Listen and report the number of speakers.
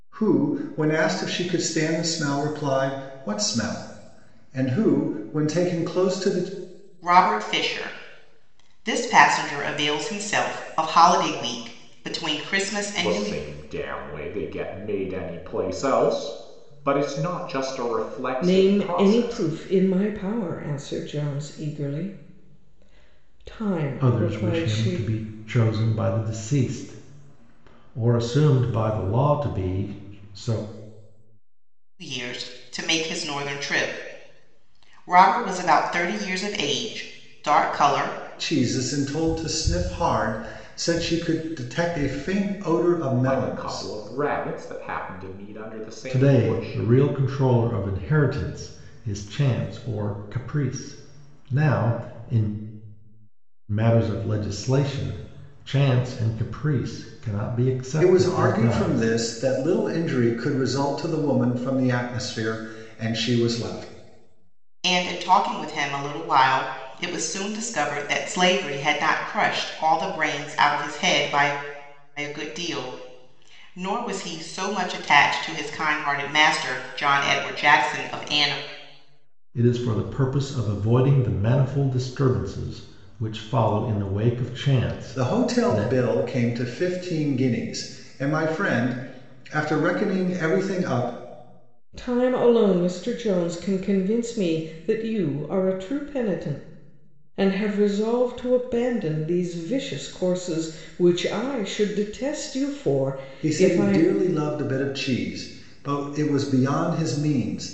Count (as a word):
five